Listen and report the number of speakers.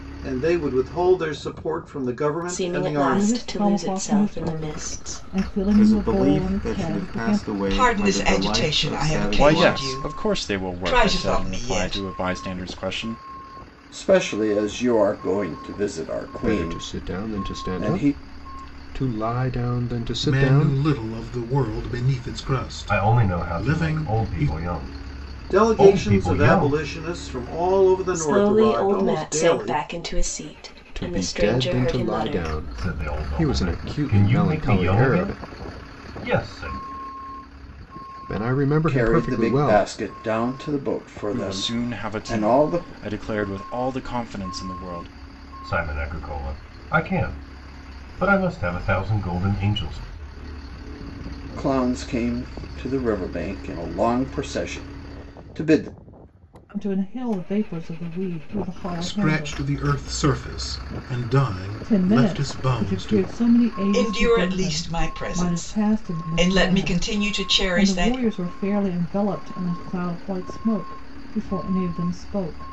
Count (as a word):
ten